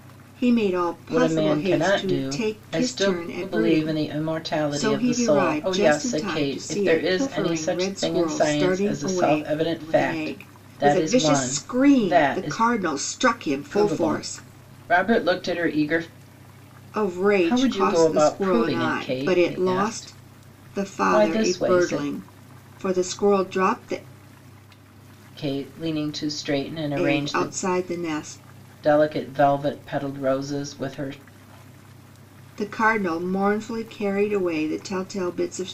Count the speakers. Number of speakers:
2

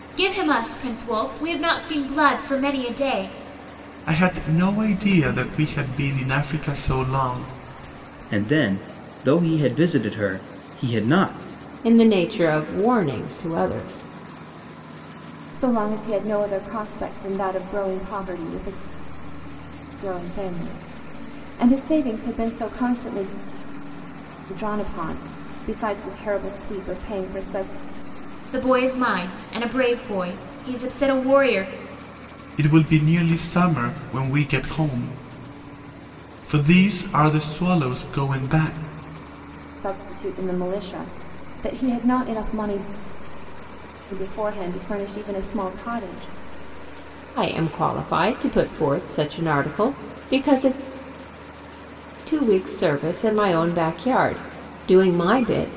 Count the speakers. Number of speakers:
5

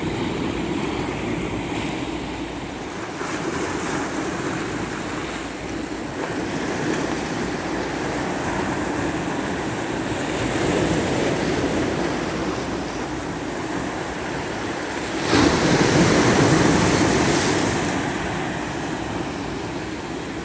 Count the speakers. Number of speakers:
0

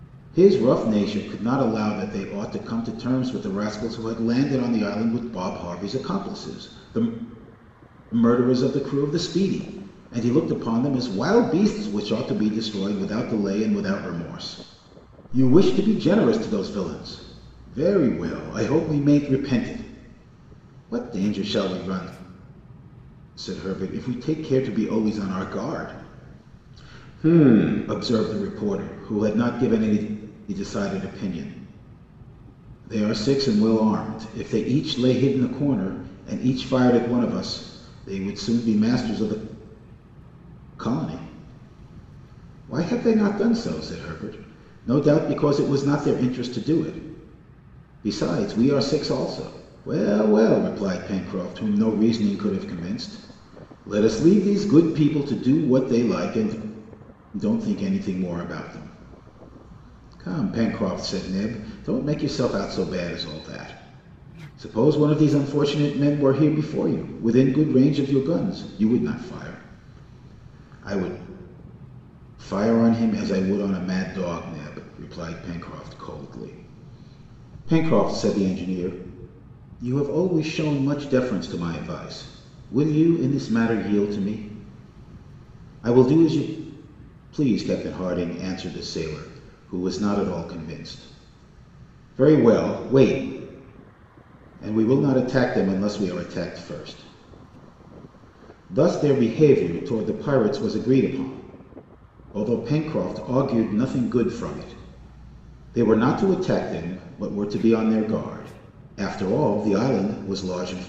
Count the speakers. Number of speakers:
1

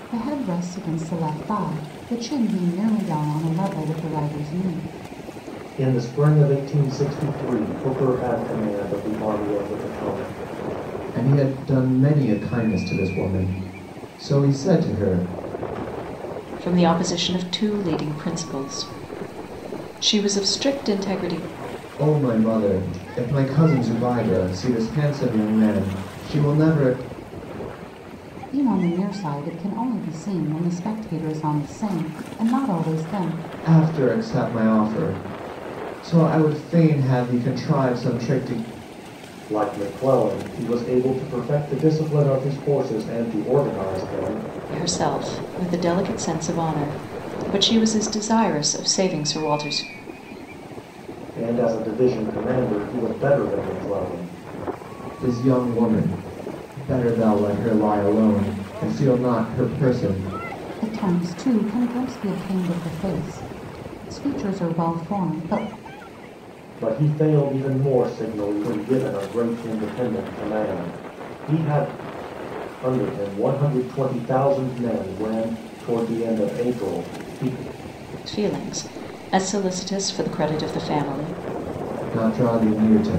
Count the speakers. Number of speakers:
4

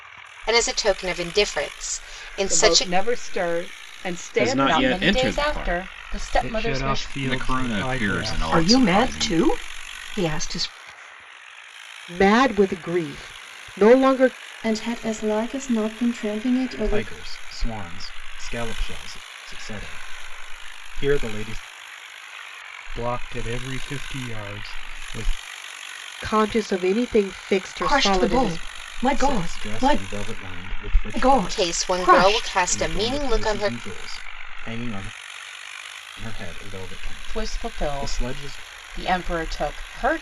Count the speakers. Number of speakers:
10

